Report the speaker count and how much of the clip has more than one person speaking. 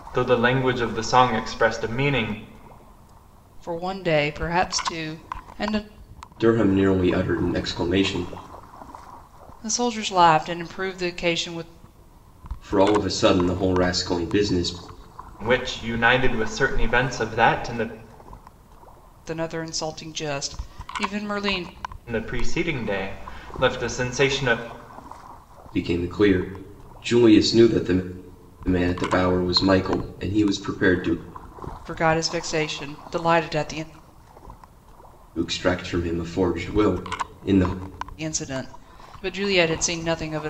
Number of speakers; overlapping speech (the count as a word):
three, no overlap